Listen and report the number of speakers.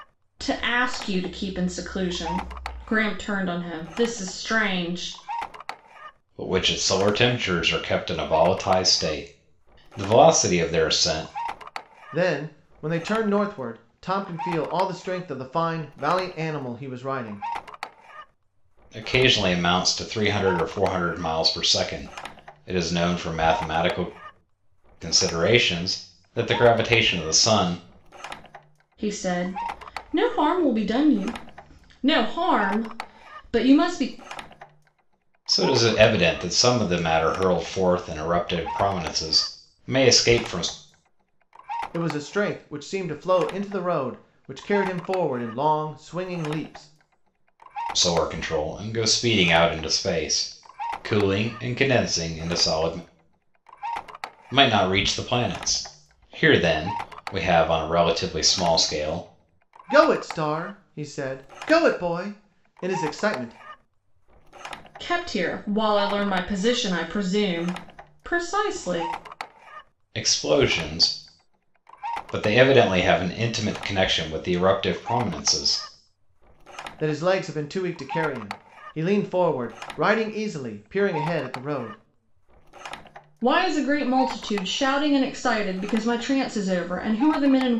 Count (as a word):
three